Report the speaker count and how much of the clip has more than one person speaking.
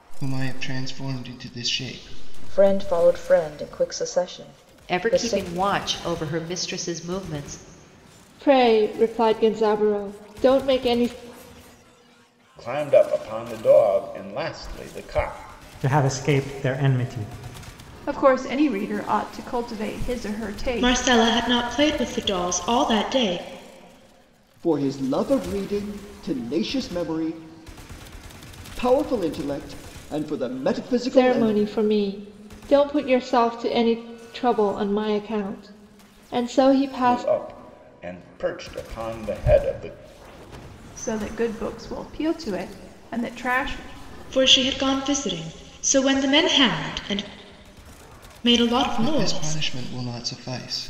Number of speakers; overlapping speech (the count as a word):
nine, about 5%